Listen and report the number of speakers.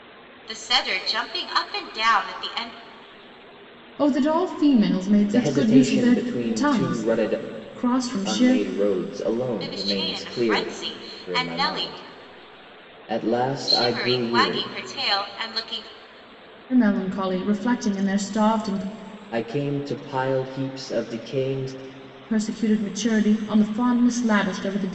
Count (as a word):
three